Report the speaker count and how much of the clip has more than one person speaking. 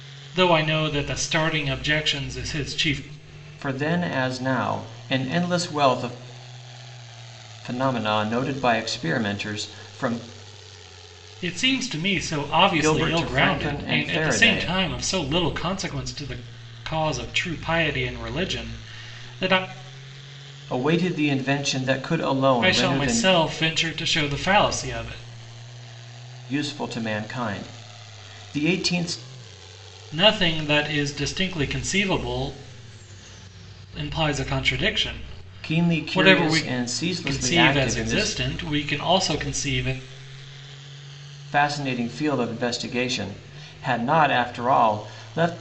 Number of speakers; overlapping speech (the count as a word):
two, about 11%